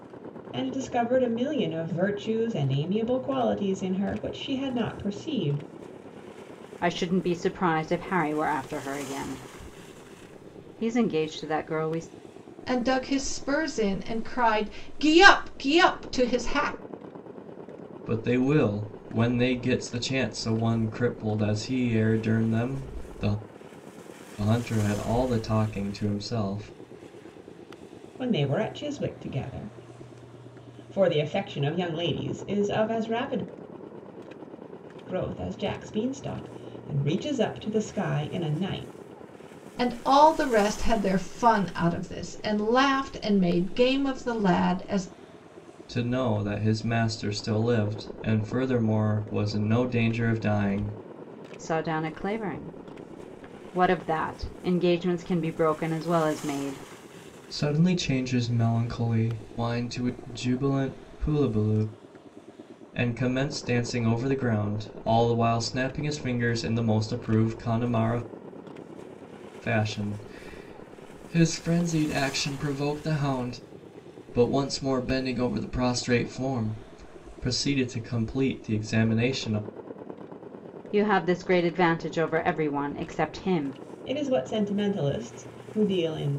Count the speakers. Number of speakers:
4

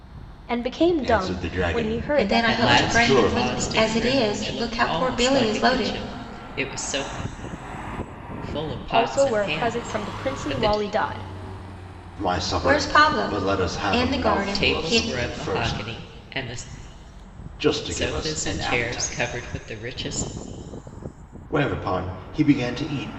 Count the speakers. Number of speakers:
4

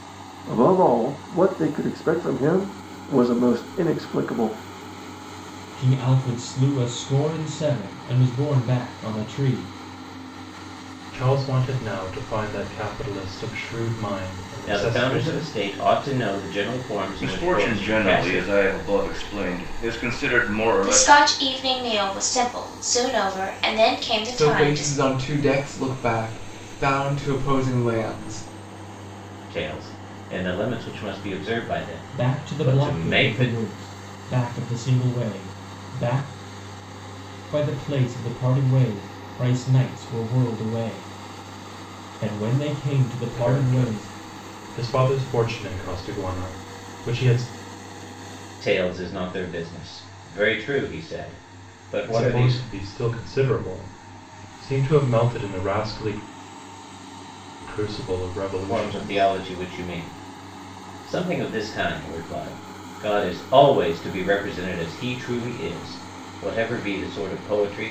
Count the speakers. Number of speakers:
7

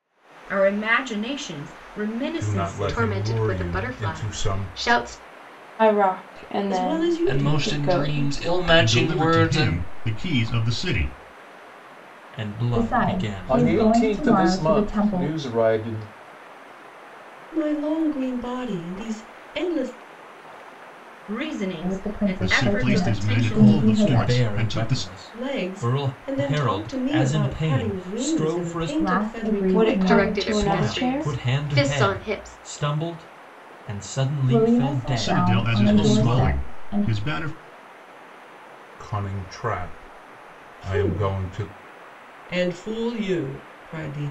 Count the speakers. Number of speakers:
10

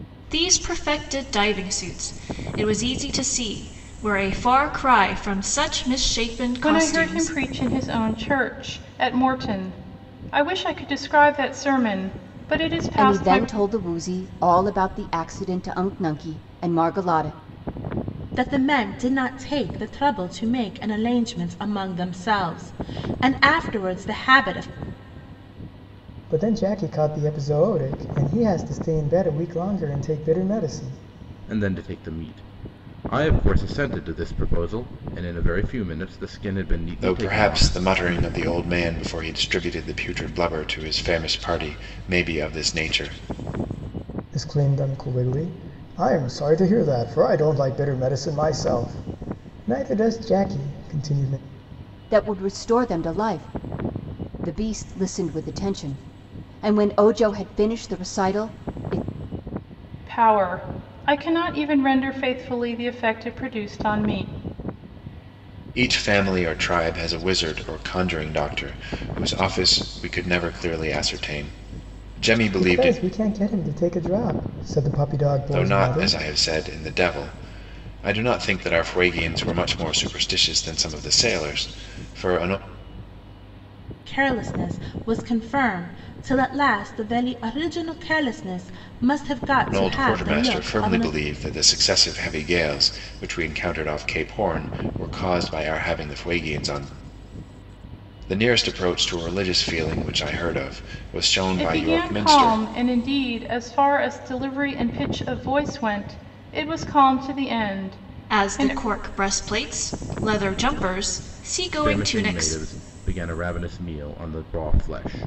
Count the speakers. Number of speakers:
7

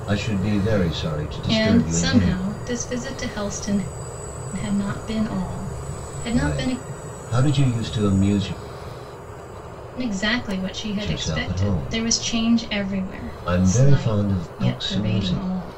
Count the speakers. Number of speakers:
2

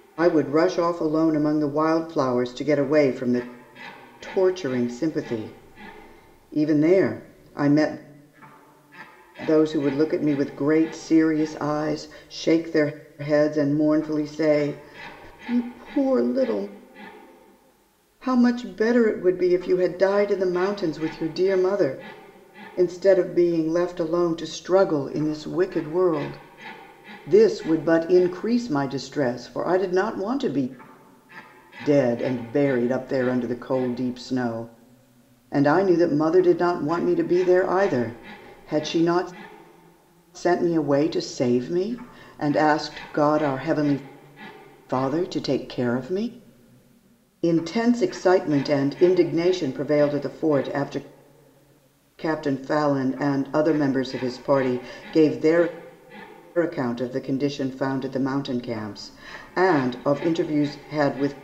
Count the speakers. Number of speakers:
1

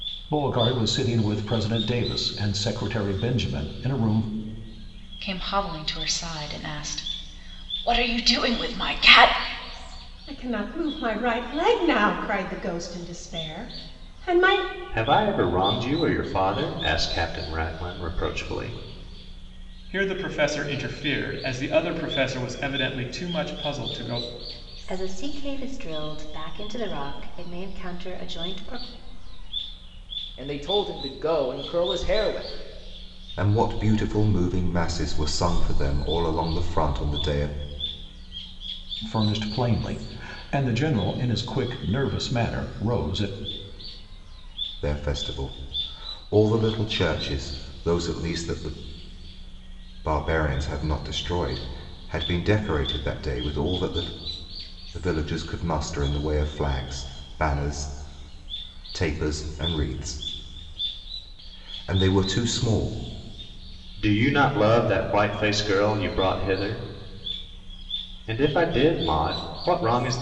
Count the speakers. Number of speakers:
8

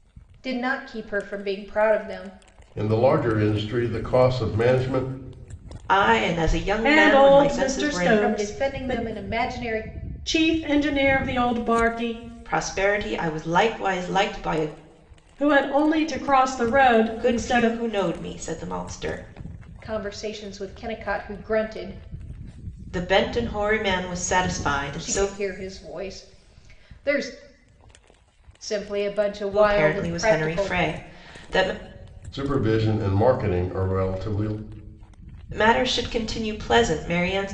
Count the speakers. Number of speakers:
4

